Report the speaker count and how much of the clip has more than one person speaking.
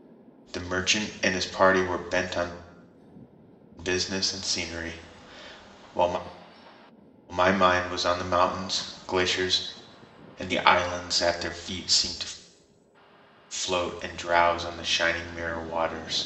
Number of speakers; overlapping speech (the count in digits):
1, no overlap